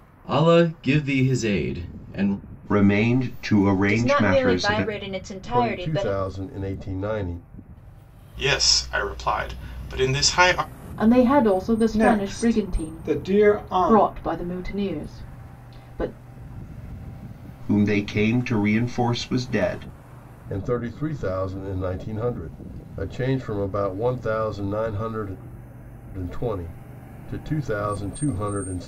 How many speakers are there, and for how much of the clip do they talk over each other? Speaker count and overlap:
seven, about 12%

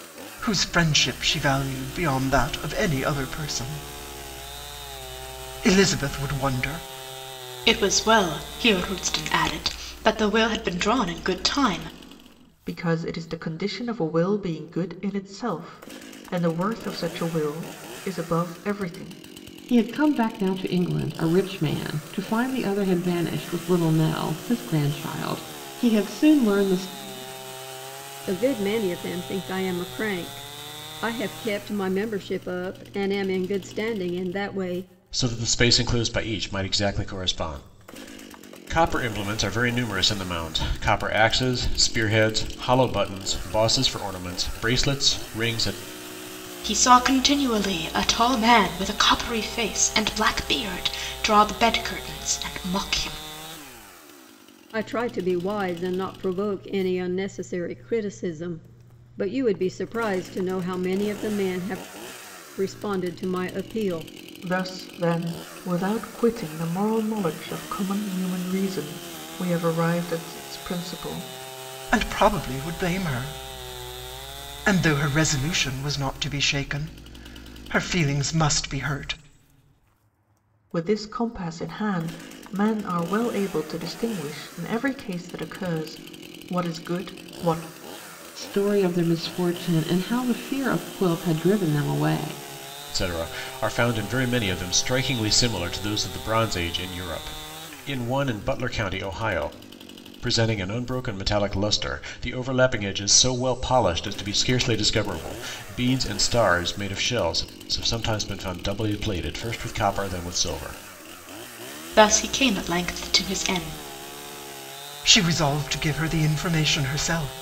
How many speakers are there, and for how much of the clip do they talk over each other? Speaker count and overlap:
six, no overlap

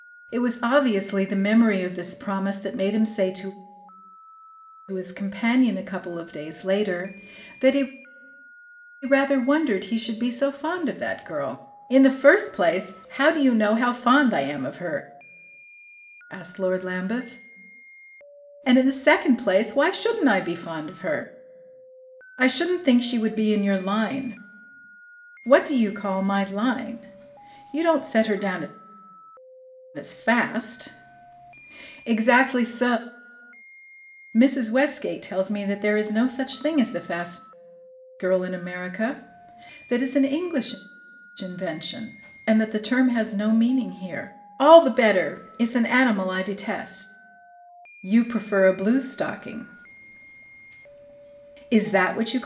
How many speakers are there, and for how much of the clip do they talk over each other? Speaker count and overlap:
one, no overlap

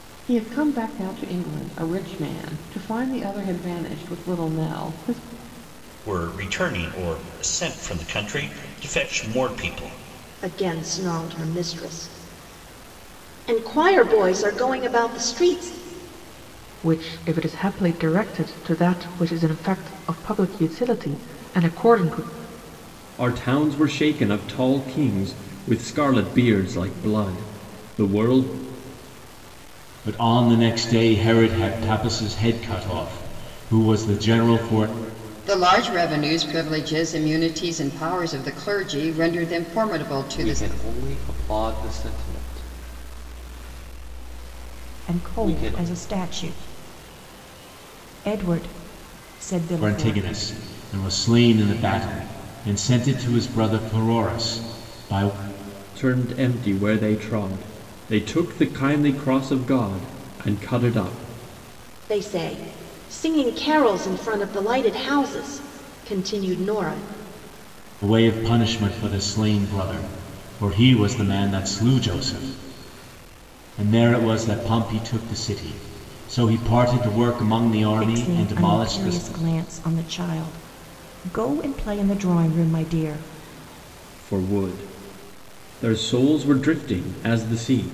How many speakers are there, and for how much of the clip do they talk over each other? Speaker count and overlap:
nine, about 3%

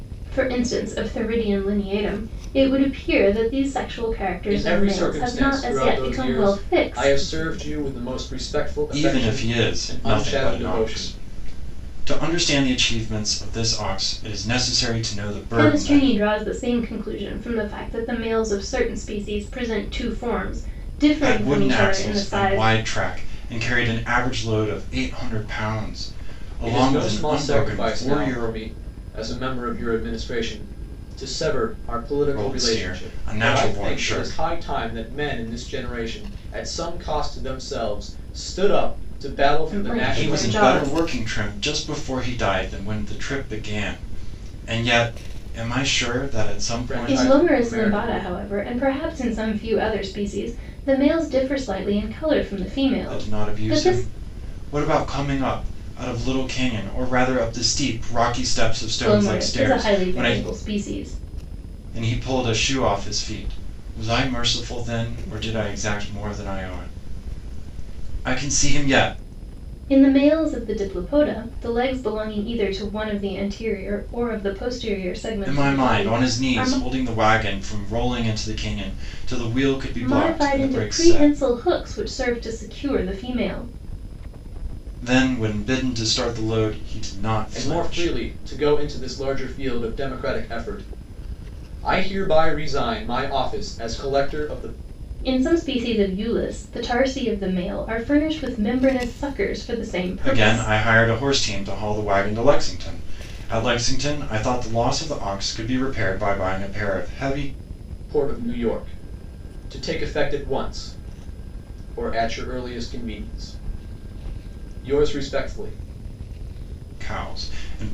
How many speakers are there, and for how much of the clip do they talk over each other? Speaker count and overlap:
three, about 17%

